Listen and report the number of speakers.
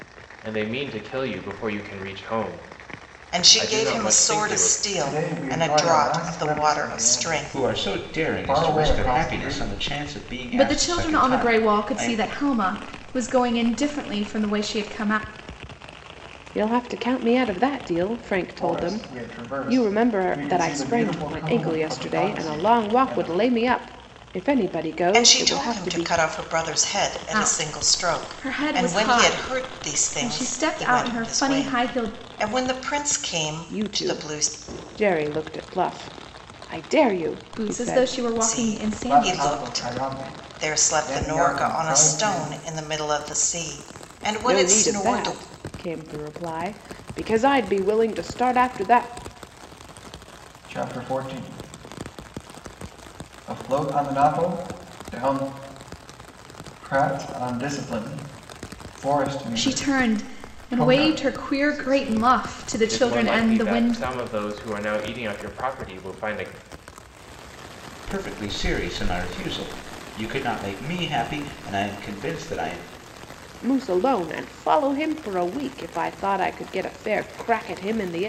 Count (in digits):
6